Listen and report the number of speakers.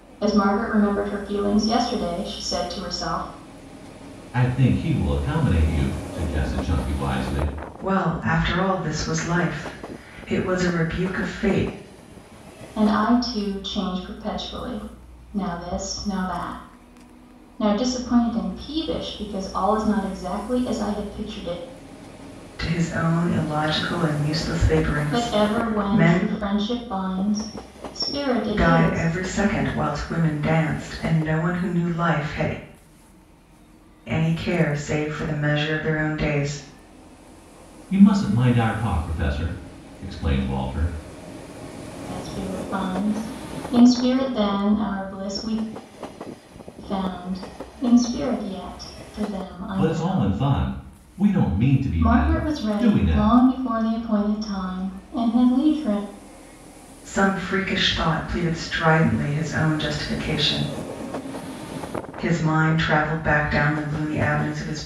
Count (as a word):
three